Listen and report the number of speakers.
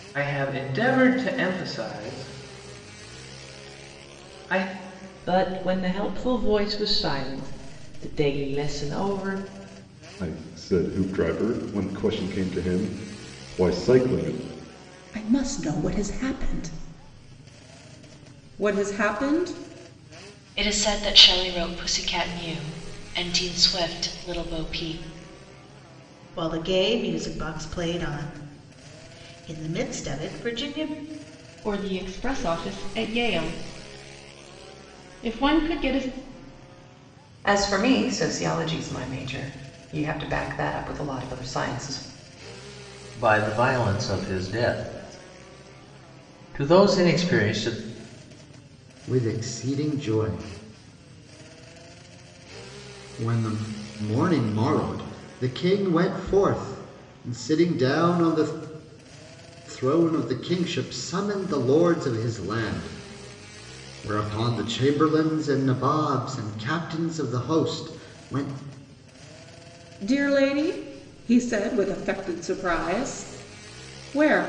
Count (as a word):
ten